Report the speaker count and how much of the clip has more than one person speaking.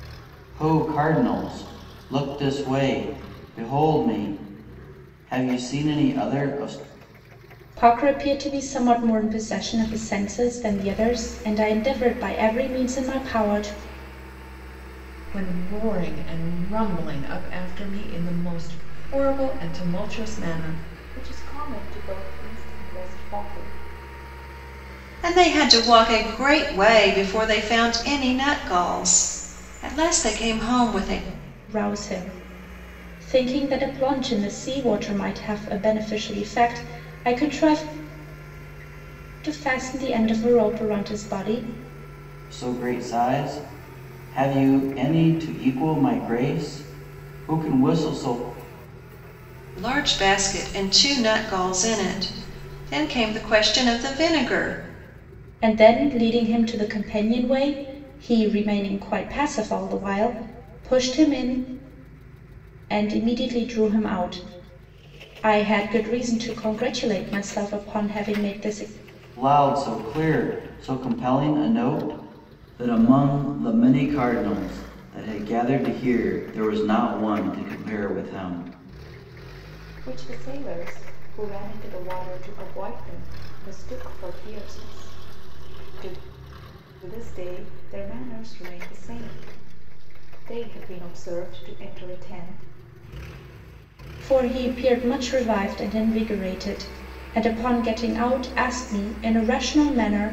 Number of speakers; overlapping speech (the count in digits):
5, no overlap